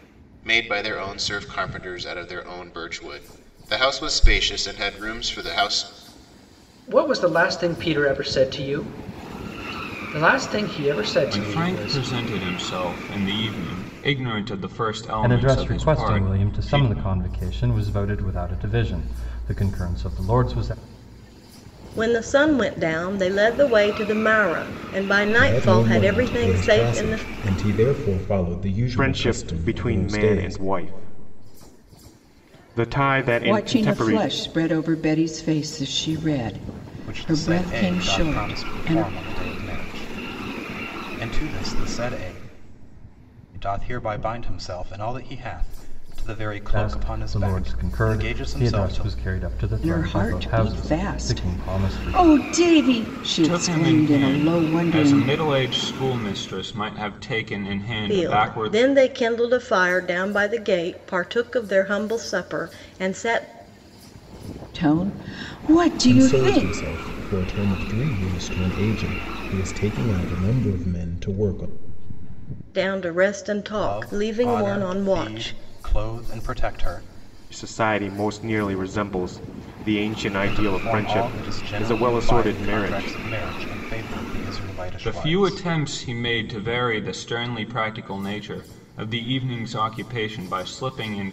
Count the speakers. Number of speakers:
nine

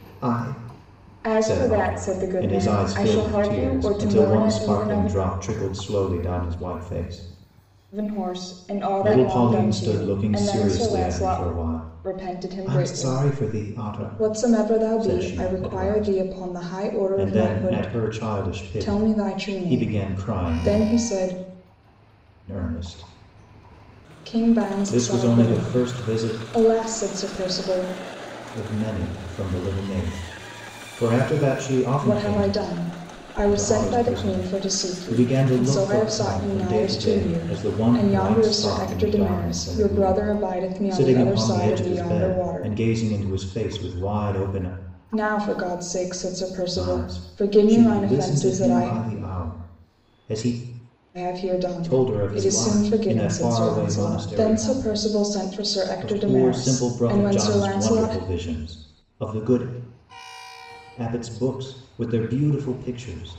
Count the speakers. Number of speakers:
two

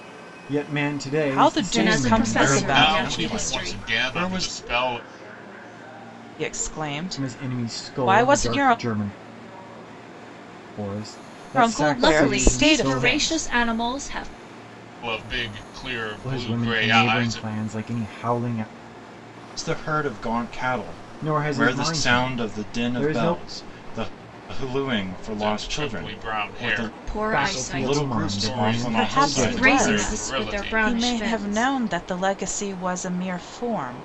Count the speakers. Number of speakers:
five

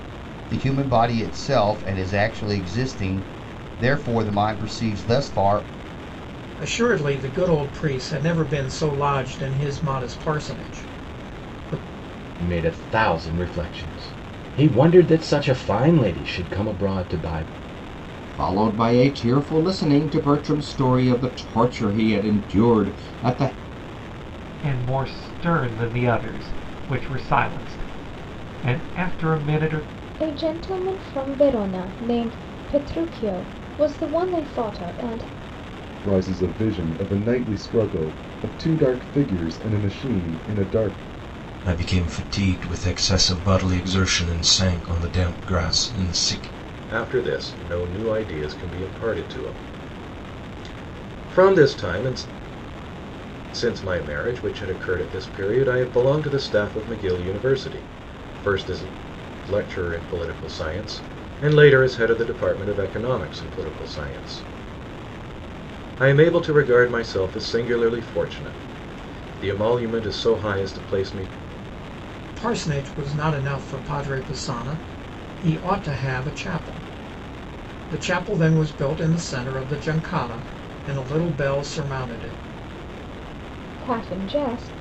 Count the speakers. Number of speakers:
nine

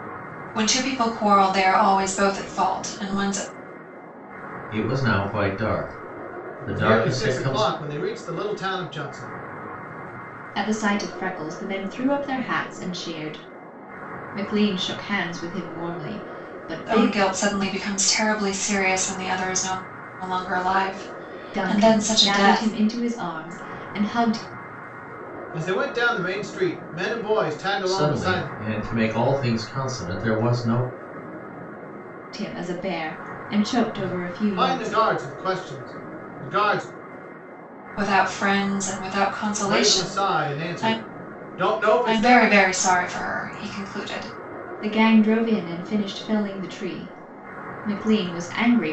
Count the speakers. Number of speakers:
four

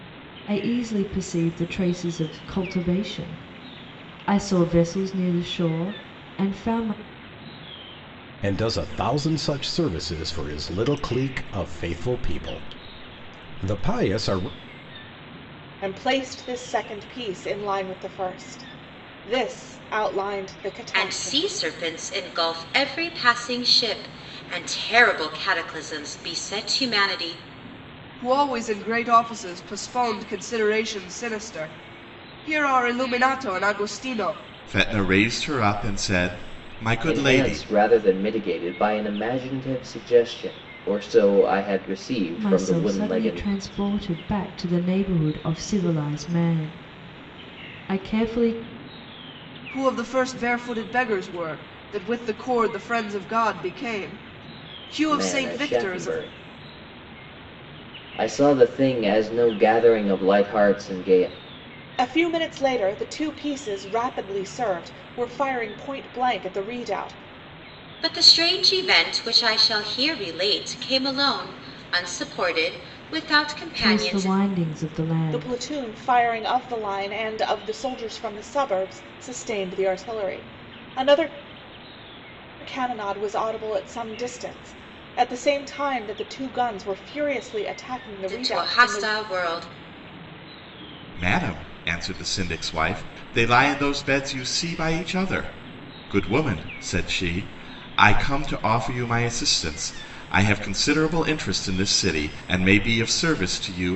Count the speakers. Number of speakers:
seven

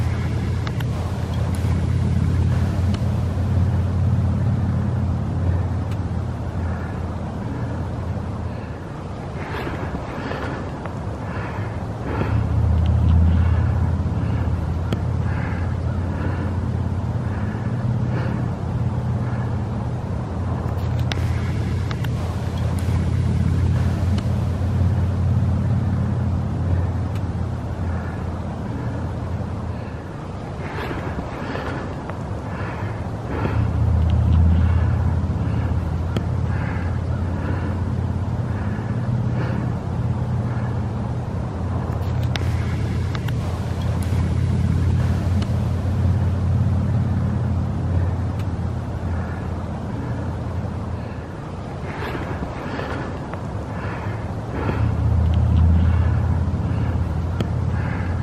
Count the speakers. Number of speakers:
zero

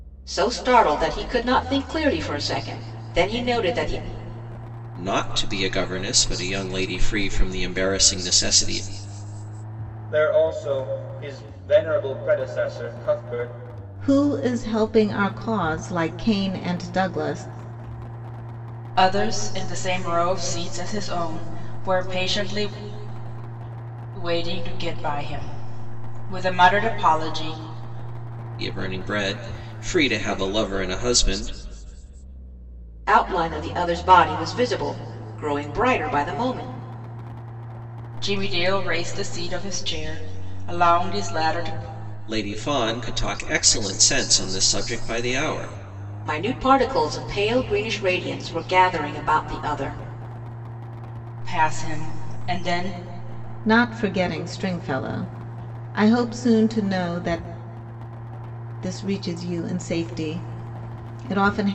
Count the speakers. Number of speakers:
five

